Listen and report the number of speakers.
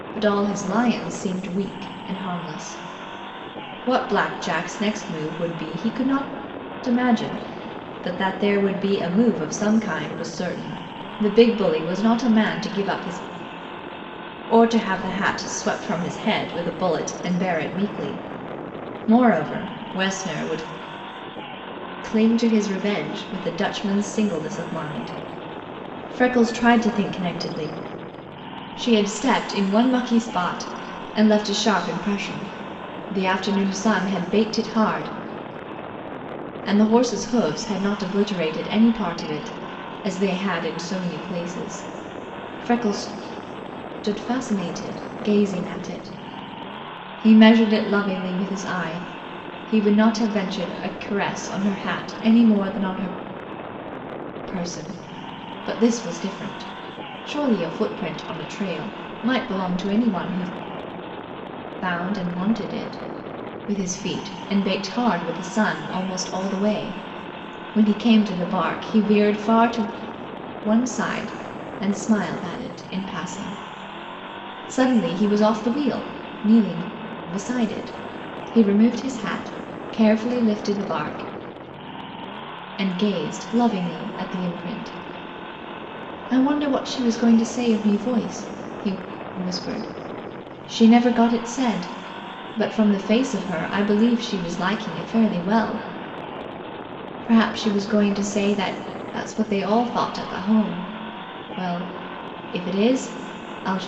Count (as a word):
one